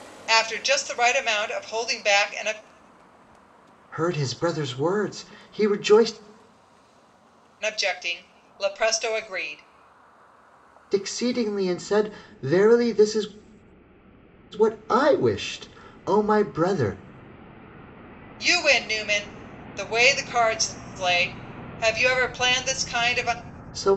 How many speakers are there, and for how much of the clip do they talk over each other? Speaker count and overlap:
2, no overlap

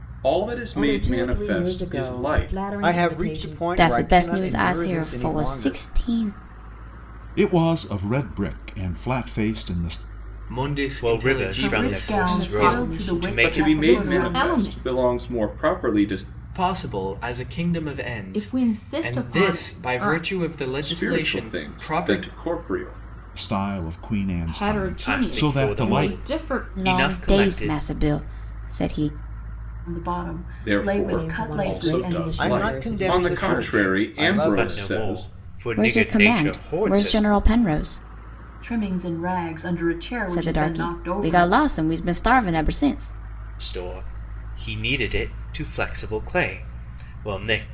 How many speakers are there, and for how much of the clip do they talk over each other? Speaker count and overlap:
9, about 48%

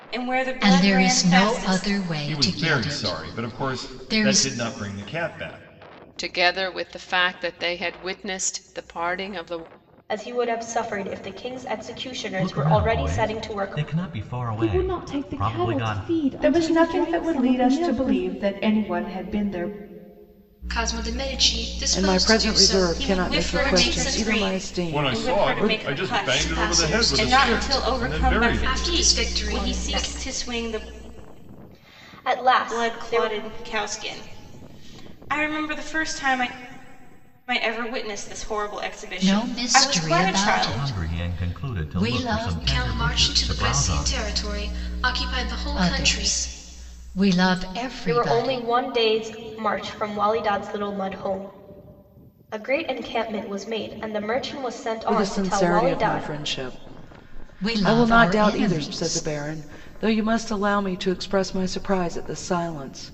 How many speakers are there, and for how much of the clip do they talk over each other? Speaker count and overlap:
10, about 43%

